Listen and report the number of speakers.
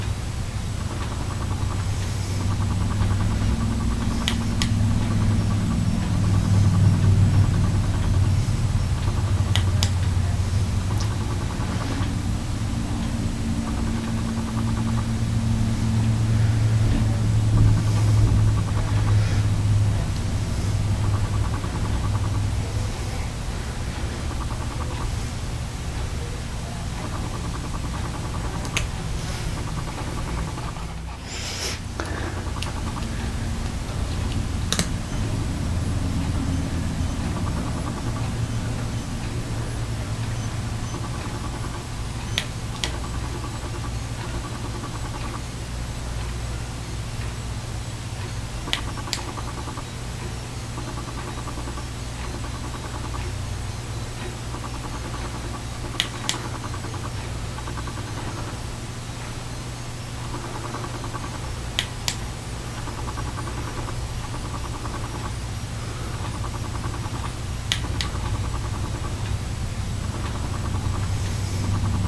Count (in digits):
0